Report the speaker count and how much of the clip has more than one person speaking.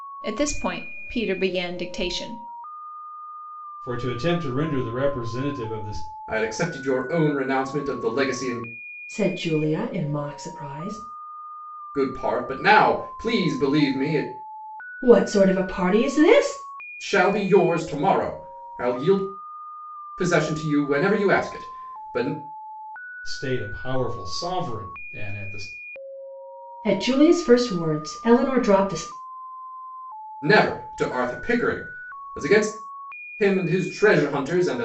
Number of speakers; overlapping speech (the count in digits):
4, no overlap